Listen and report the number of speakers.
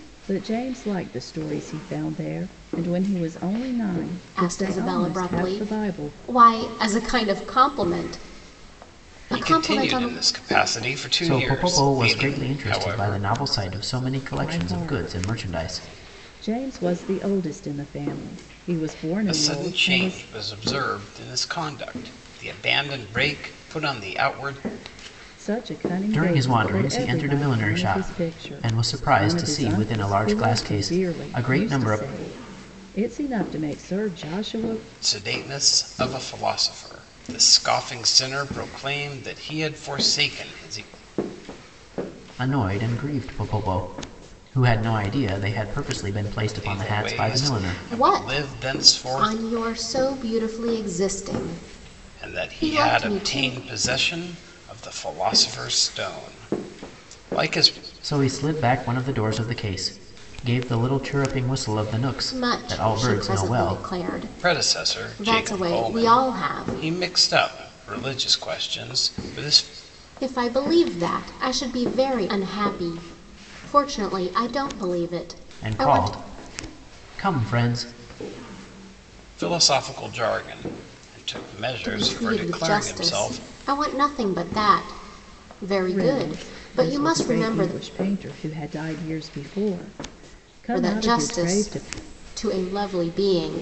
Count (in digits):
4